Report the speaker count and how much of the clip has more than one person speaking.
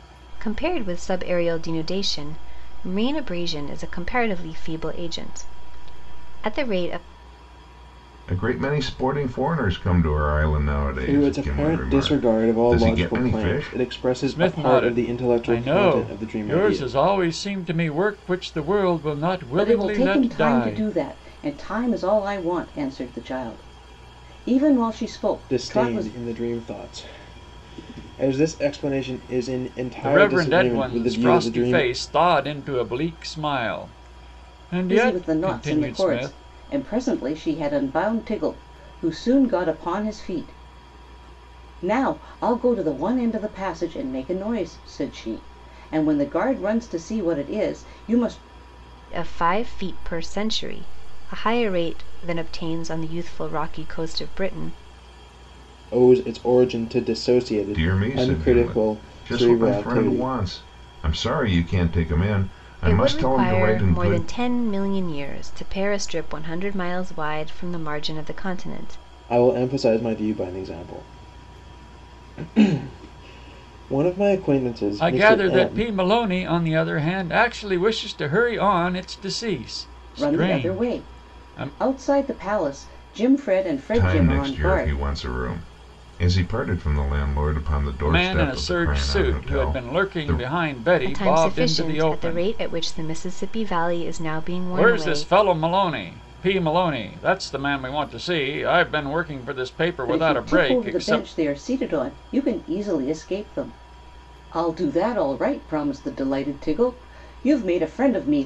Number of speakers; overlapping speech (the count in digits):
5, about 23%